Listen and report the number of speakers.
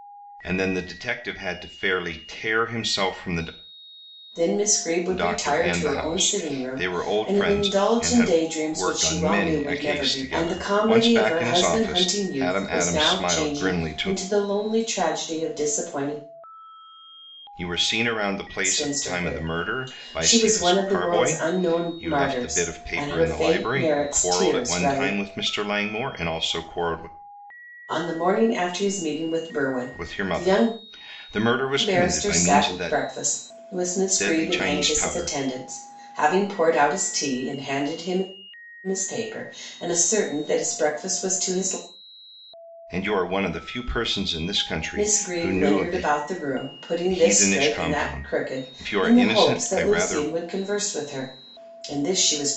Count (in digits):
2